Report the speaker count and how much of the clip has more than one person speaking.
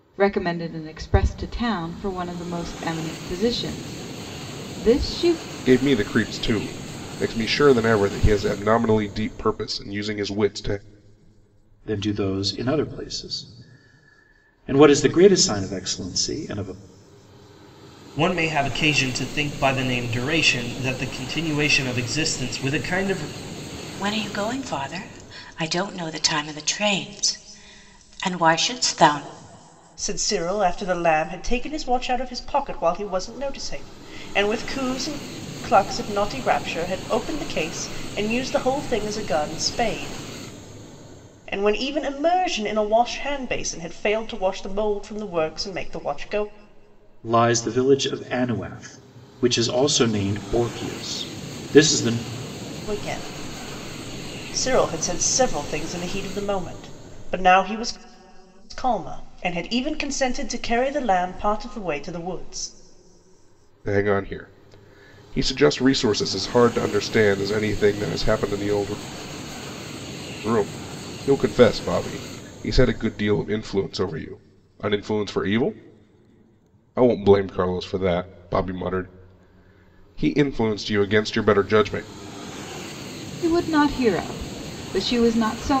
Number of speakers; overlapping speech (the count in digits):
6, no overlap